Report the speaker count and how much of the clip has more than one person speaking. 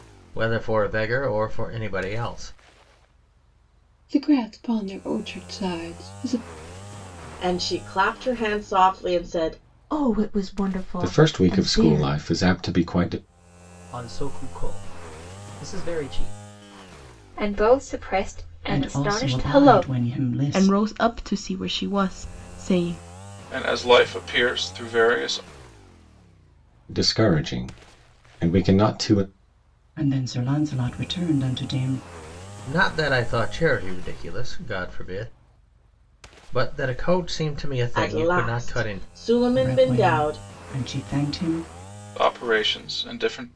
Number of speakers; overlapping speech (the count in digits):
10, about 11%